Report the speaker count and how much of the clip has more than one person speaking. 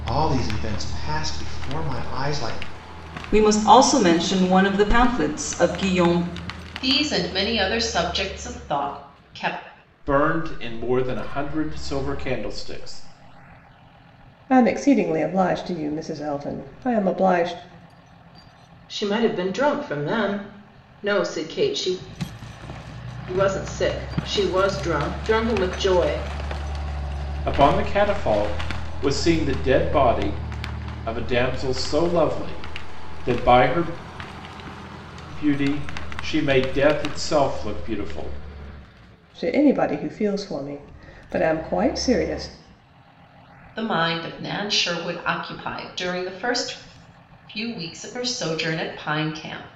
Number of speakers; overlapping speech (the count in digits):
6, no overlap